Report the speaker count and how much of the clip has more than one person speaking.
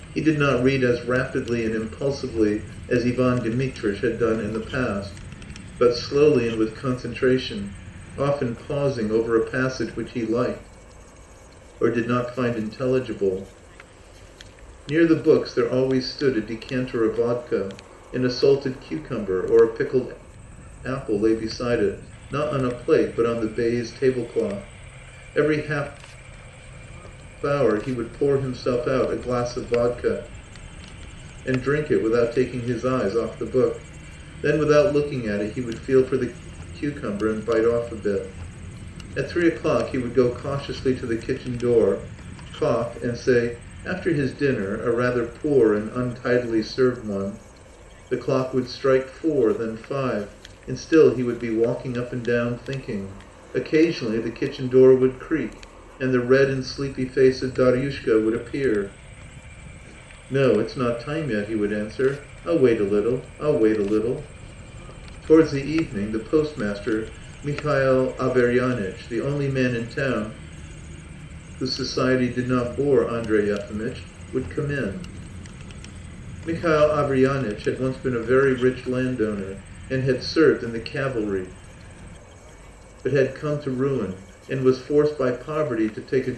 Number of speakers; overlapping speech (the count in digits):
1, no overlap